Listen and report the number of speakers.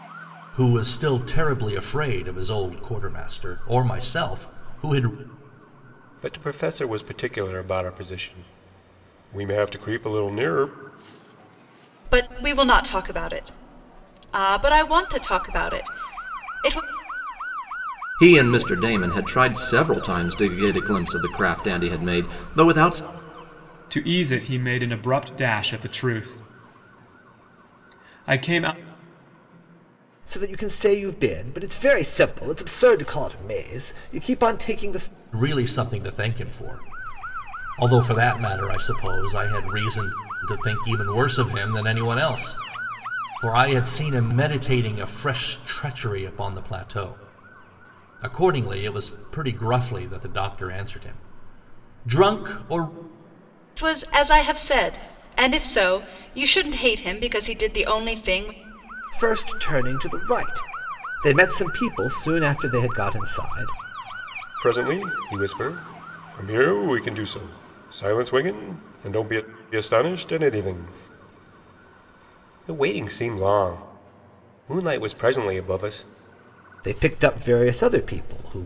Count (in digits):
6